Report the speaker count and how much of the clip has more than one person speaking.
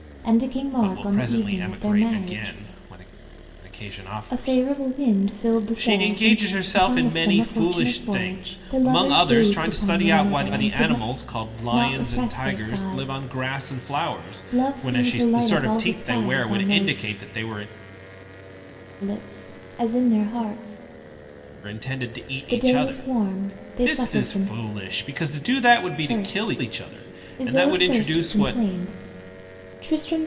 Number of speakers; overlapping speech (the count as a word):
two, about 56%